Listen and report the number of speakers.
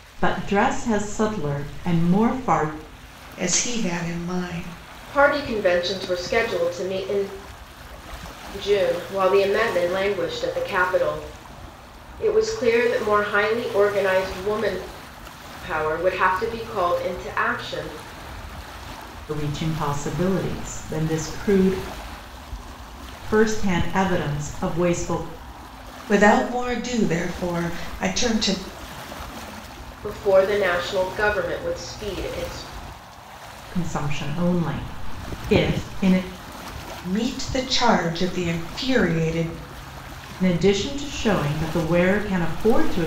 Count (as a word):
three